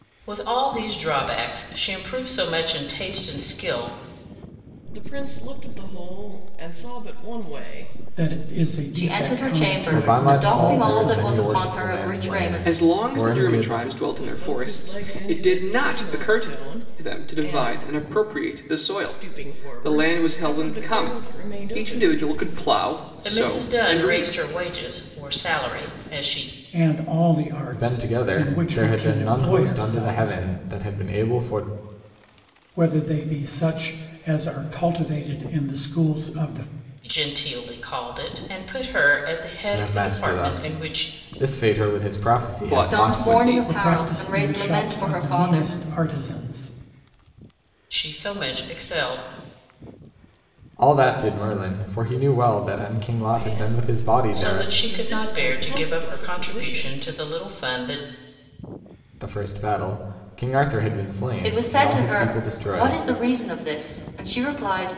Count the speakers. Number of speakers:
six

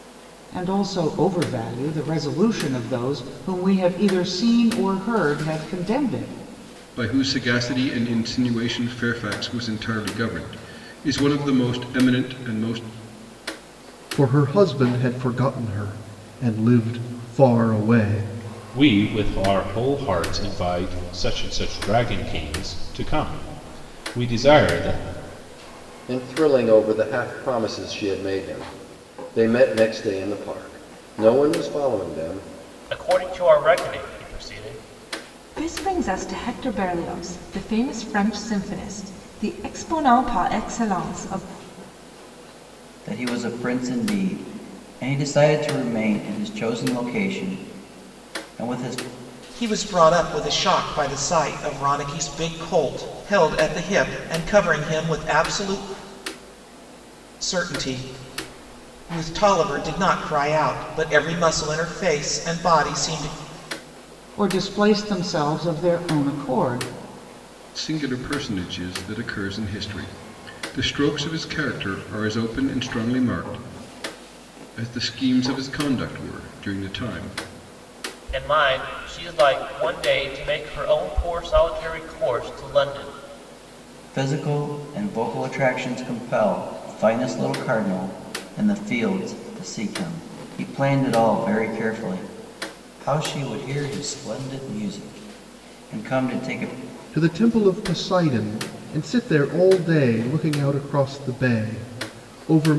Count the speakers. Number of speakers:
nine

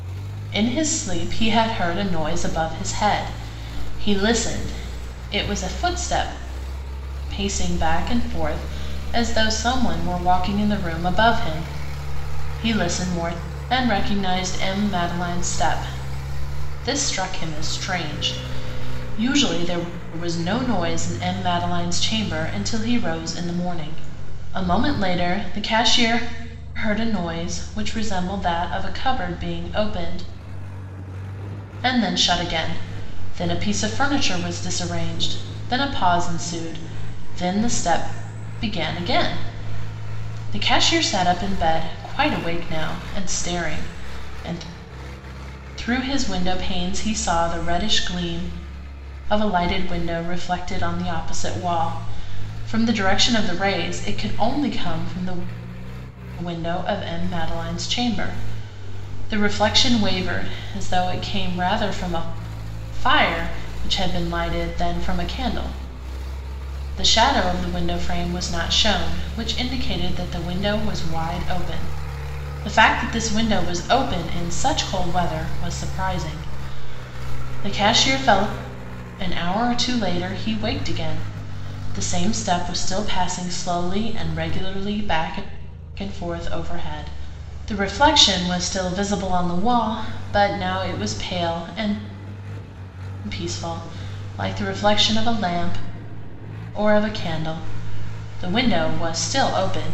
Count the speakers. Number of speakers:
one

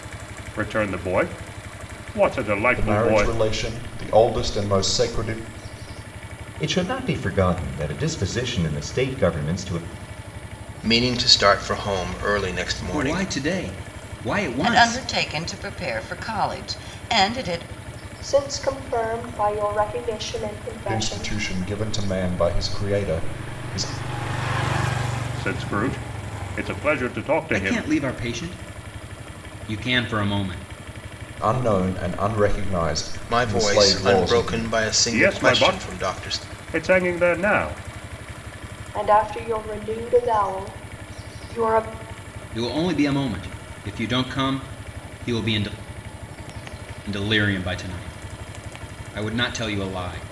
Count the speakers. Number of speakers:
seven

